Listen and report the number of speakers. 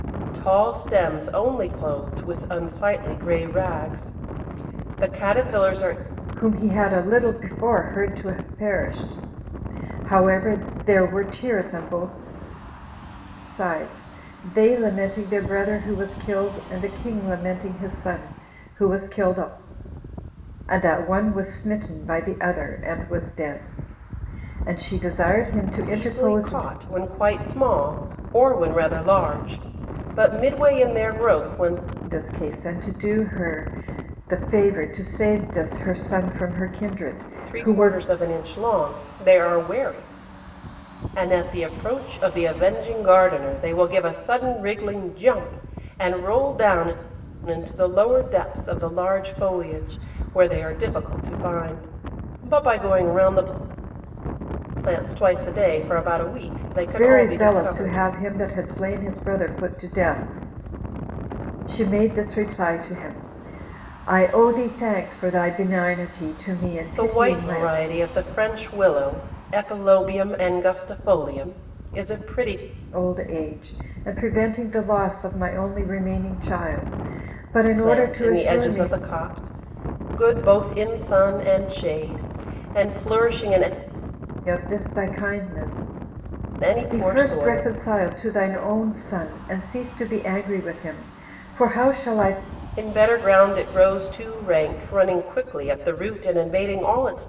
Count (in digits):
2